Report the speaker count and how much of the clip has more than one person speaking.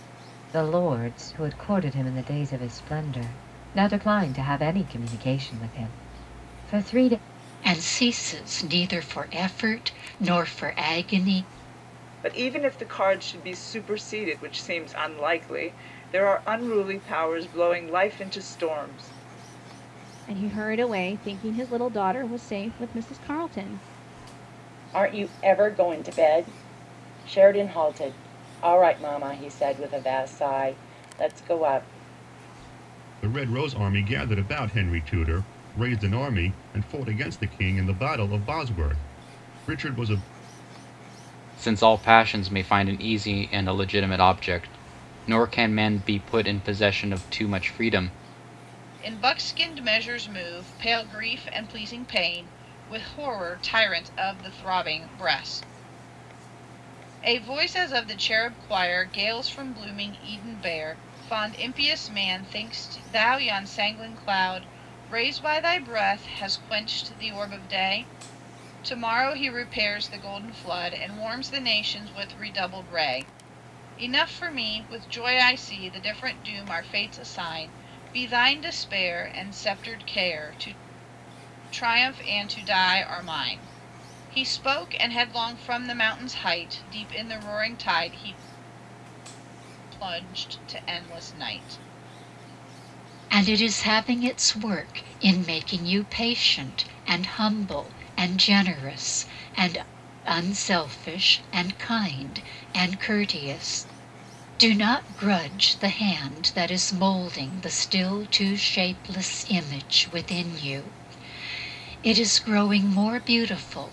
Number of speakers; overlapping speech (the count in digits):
8, no overlap